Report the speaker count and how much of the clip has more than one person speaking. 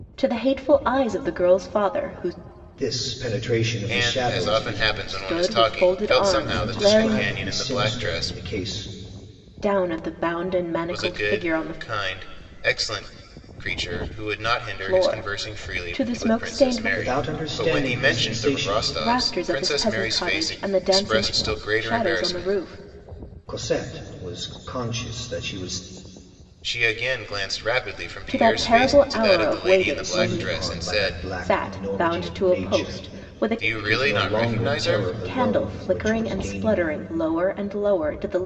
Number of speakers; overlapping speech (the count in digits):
3, about 54%